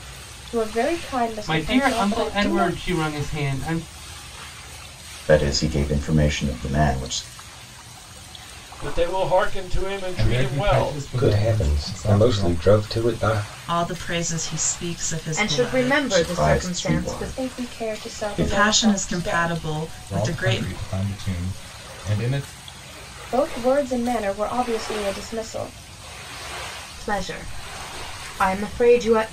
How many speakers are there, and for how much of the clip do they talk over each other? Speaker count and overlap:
8, about 29%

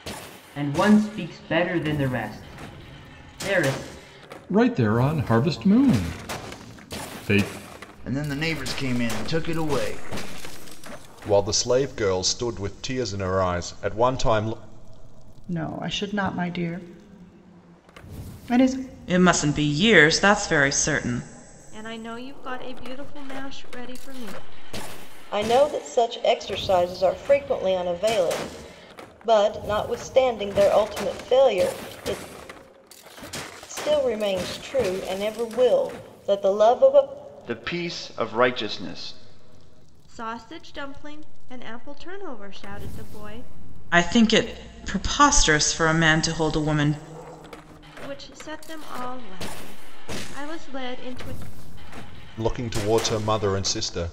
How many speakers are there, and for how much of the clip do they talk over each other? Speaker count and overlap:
8, no overlap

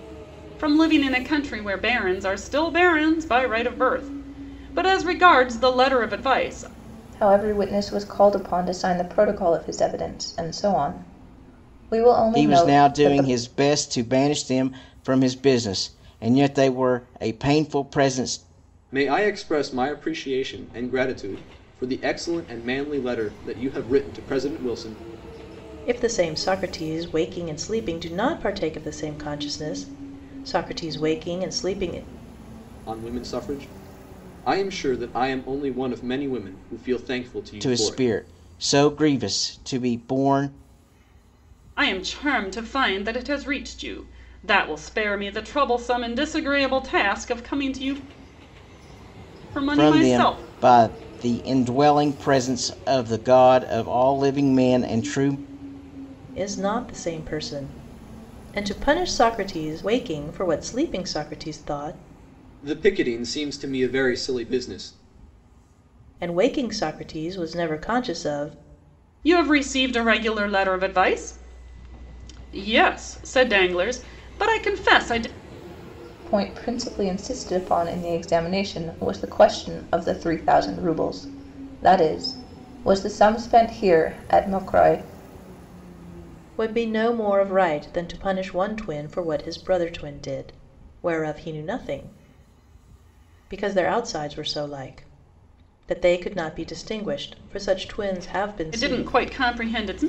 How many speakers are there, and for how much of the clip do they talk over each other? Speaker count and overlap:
5, about 3%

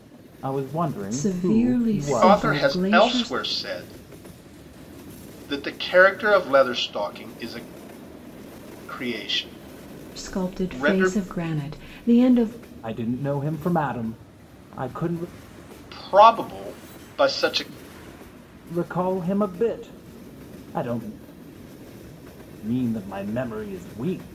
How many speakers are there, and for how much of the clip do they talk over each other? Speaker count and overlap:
3, about 13%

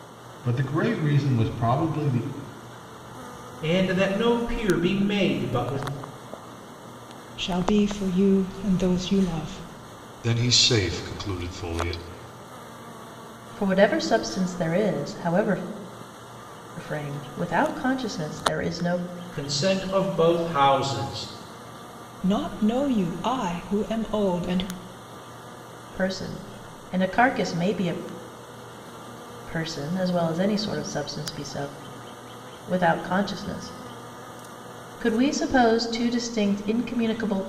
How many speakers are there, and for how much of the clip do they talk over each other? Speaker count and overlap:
5, no overlap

